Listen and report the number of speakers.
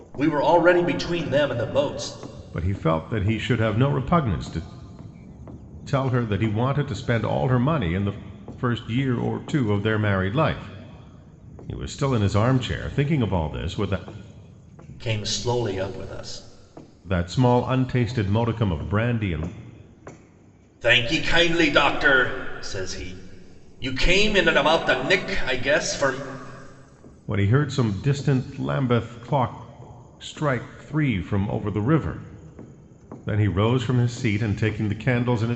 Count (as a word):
two